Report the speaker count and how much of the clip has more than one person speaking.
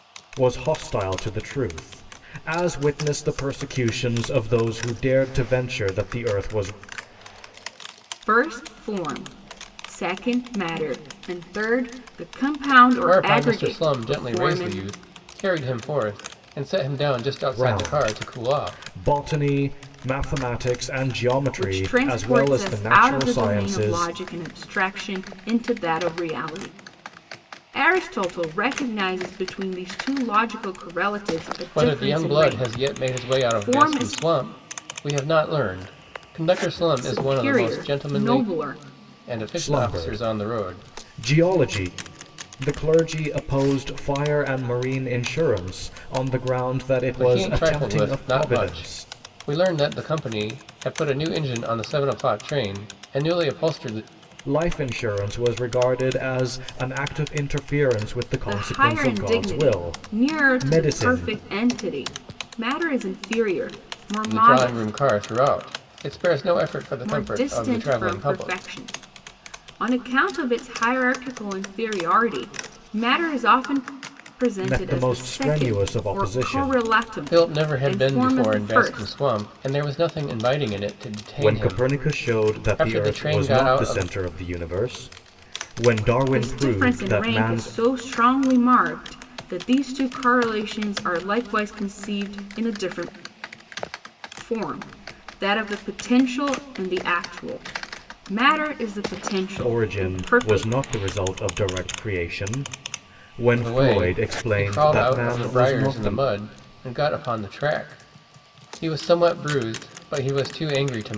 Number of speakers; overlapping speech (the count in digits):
3, about 27%